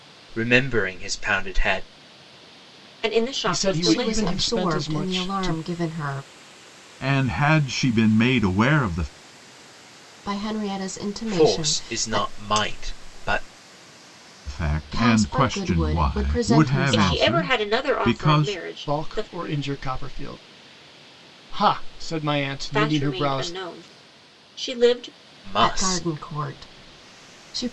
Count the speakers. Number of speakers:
5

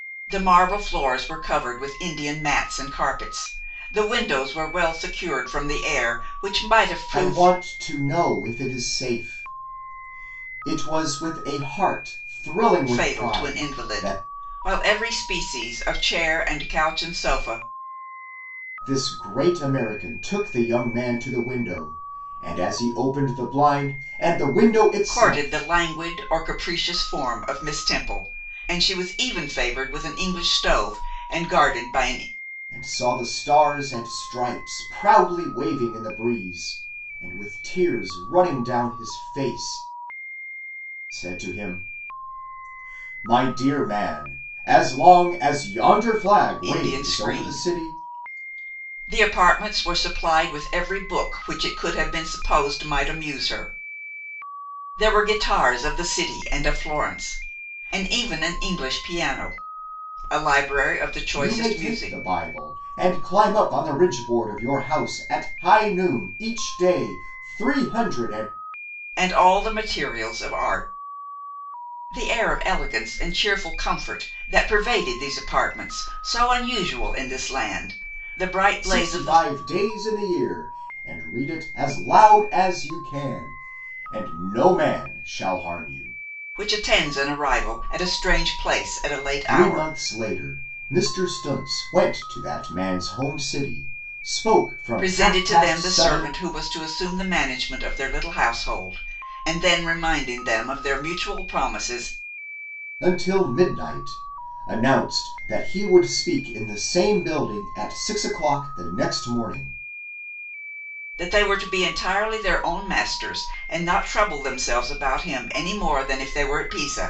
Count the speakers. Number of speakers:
2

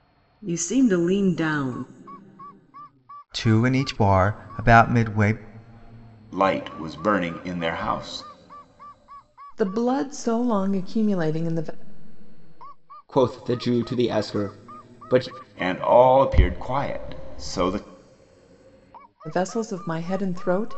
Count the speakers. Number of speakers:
5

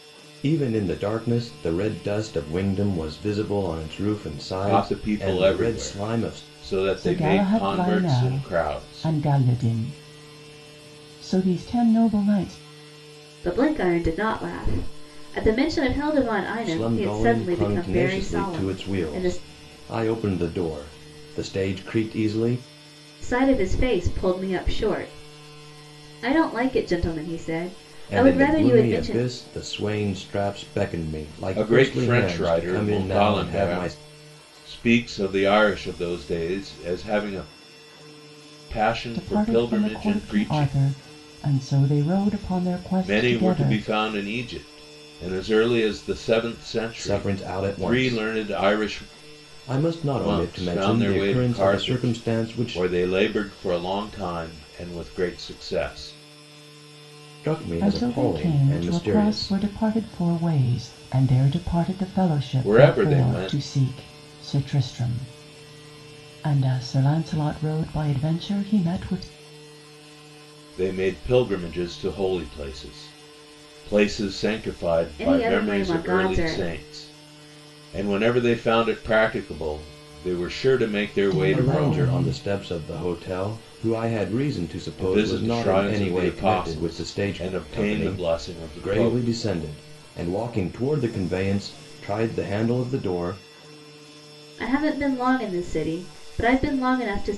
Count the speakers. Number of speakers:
4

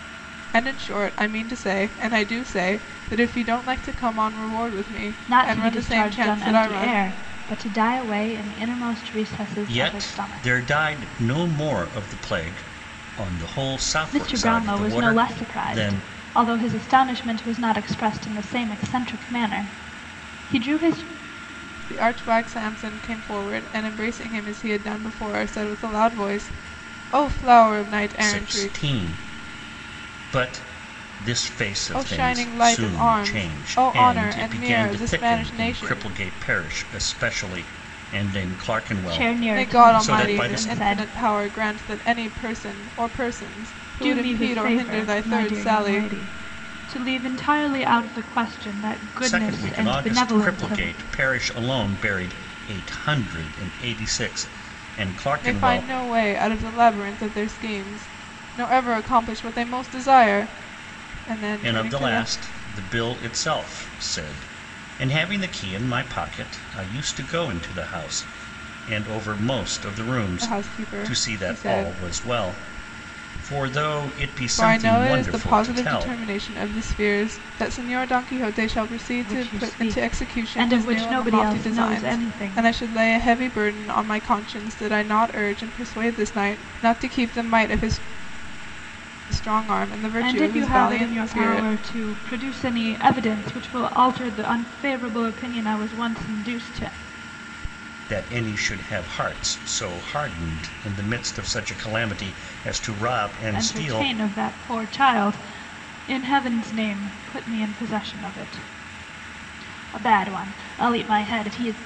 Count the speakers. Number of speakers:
3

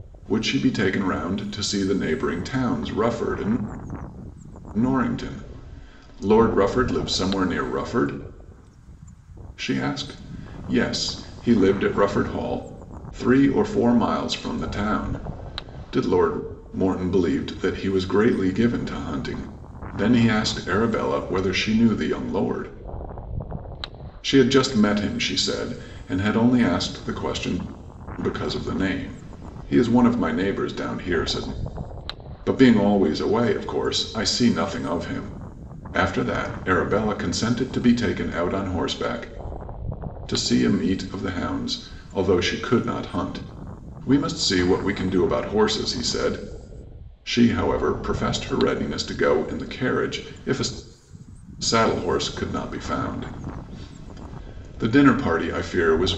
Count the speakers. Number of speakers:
1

